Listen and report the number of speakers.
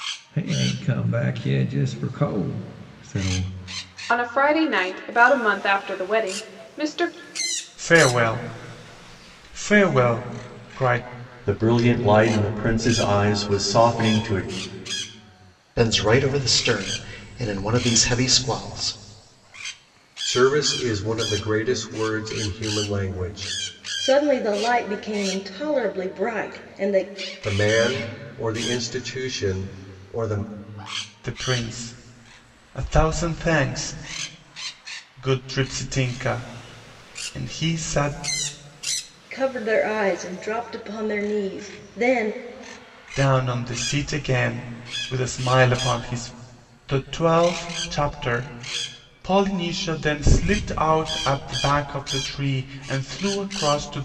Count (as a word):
seven